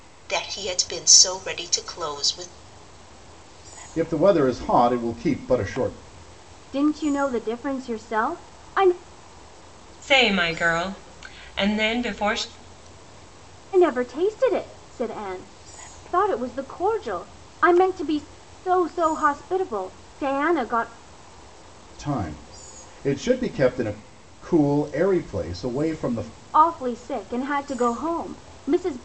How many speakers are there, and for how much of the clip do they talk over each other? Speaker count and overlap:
4, no overlap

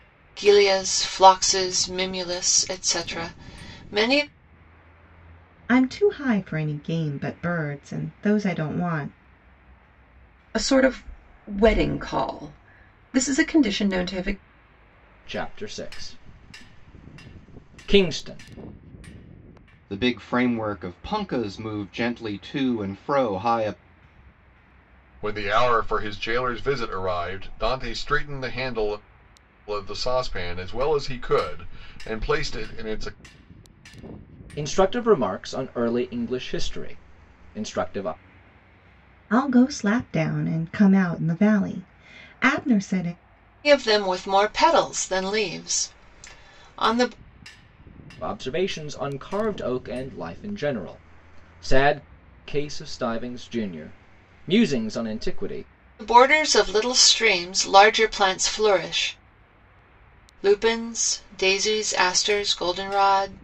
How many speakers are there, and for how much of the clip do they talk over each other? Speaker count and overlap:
6, no overlap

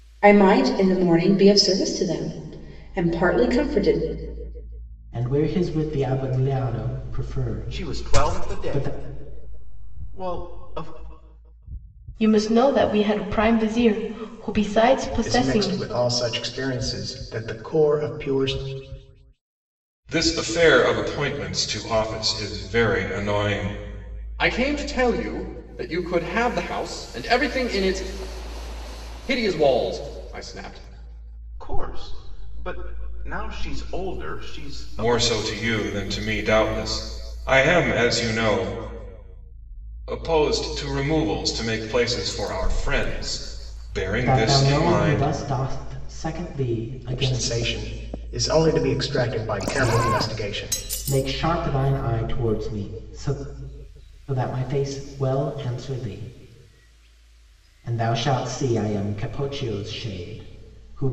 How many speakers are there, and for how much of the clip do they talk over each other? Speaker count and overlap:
7, about 8%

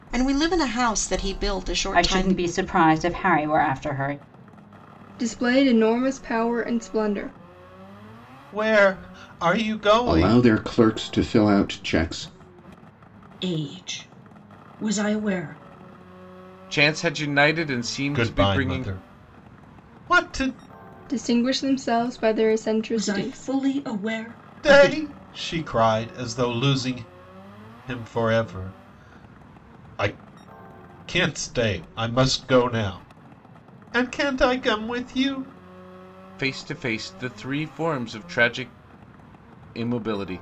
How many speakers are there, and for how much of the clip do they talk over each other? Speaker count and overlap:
7, about 7%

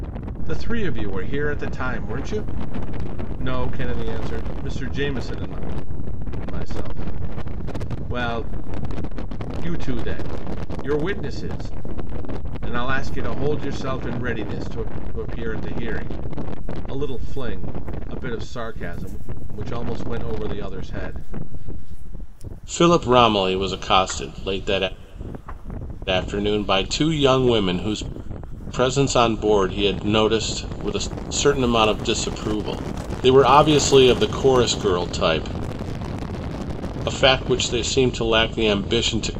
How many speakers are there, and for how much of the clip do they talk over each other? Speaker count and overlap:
1, no overlap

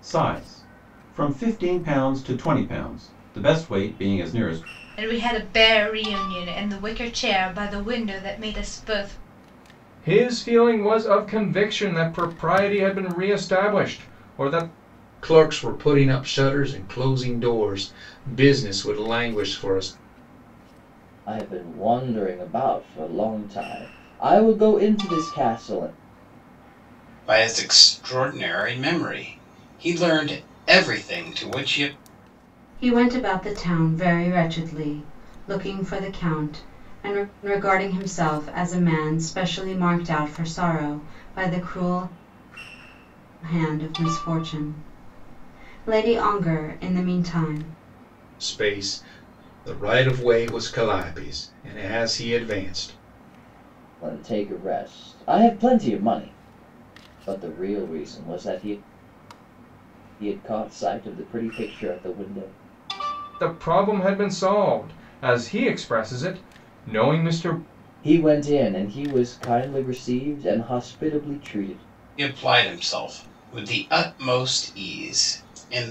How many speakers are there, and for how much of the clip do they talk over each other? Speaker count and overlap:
7, no overlap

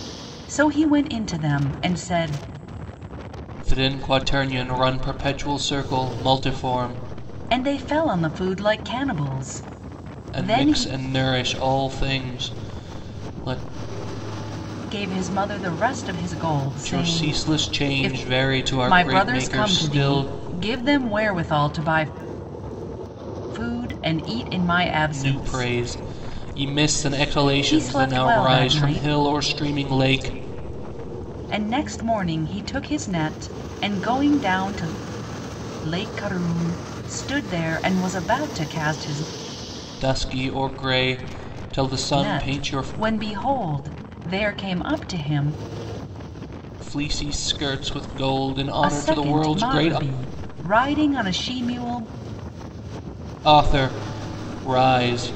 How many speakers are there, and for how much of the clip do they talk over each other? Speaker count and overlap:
2, about 14%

